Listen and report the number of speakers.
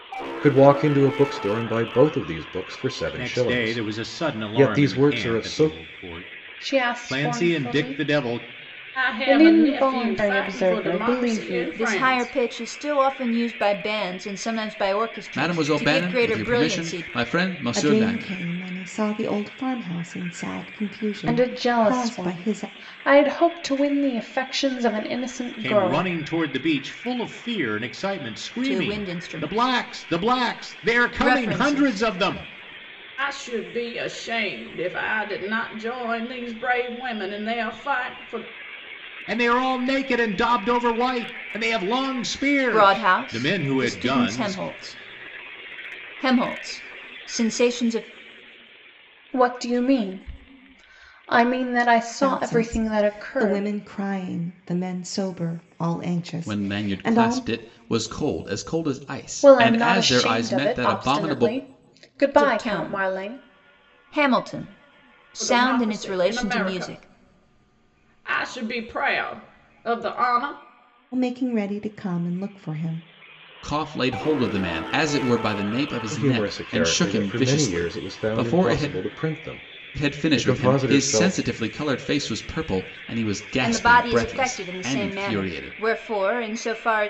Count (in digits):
7